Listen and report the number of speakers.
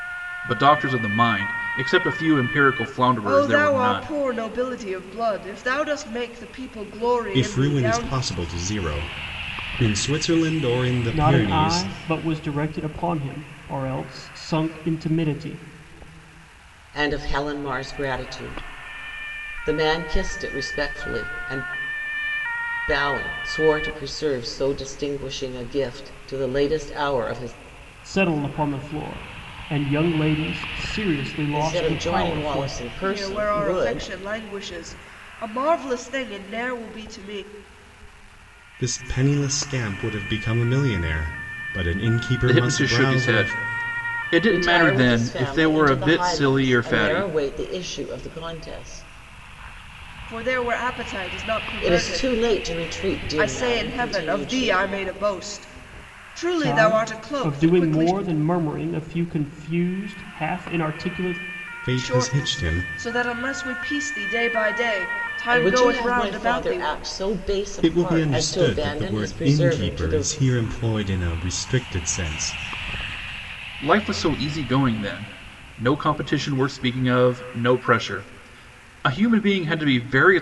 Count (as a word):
five